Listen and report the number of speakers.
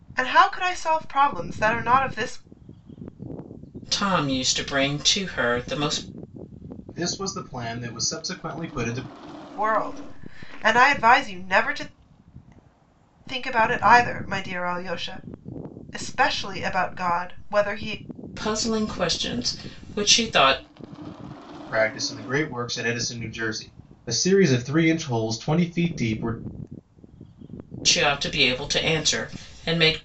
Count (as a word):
three